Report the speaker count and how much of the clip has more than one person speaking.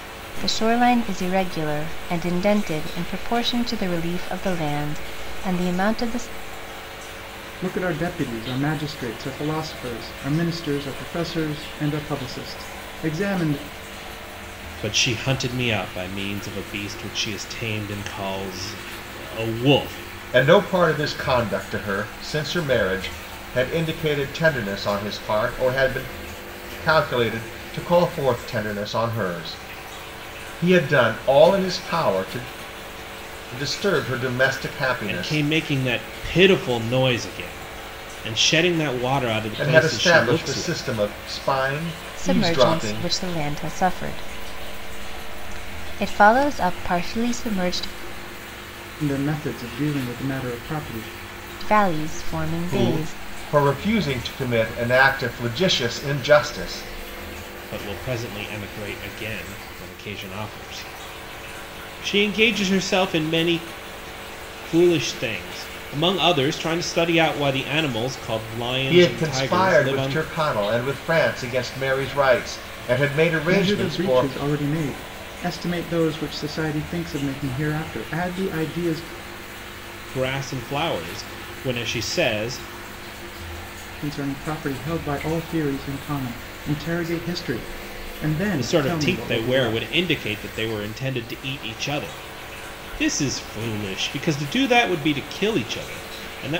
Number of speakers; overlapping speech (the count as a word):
four, about 7%